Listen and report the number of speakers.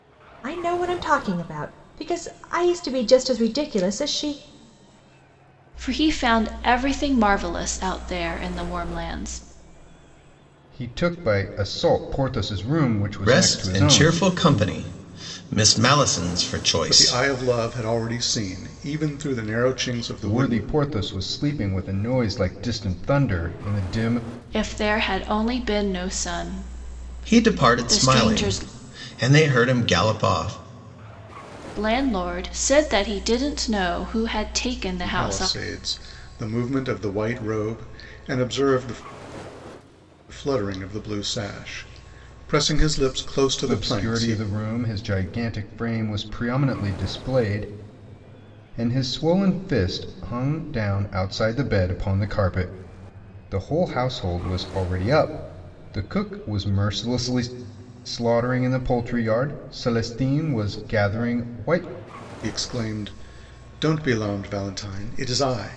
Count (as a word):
five